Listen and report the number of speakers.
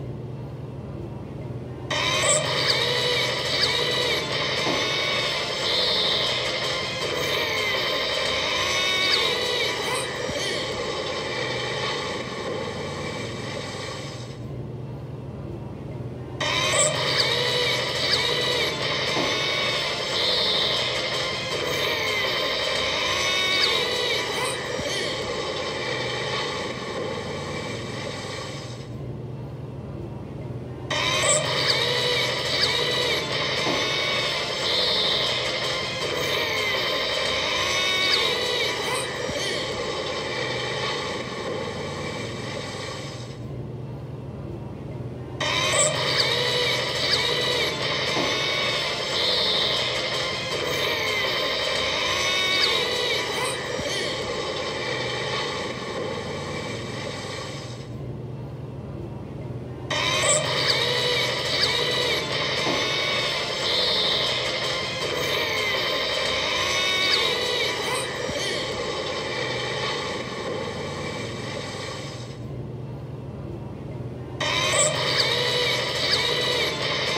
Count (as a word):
zero